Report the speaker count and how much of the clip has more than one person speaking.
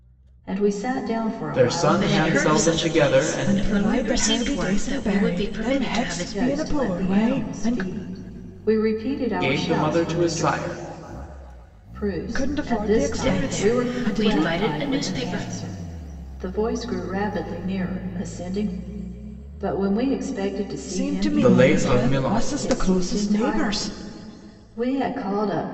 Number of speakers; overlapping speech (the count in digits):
4, about 53%